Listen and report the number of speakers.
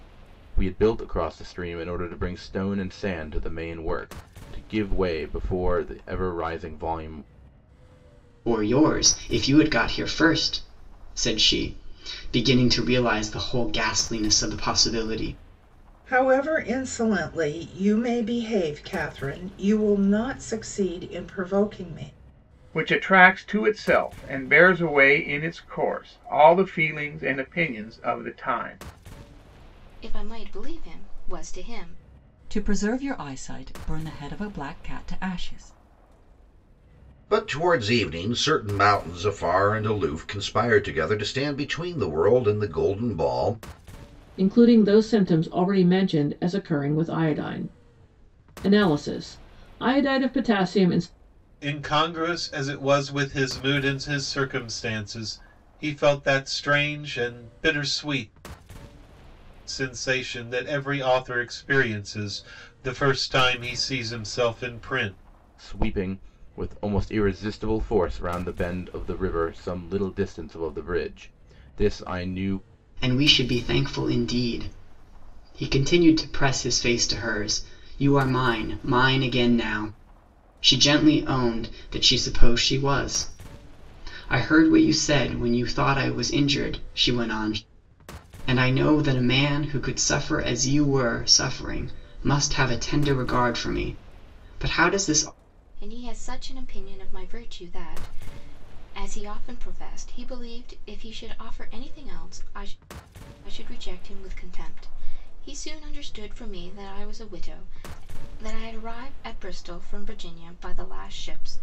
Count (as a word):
nine